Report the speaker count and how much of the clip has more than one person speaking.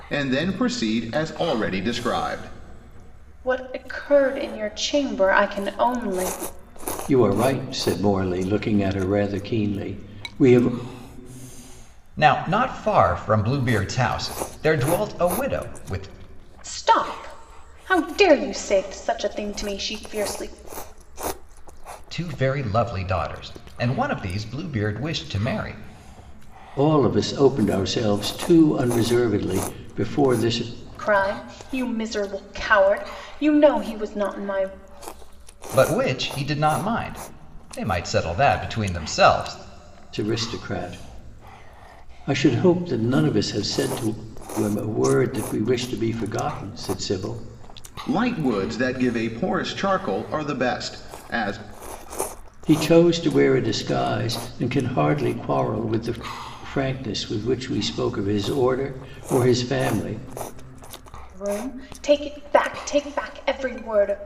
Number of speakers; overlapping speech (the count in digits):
4, no overlap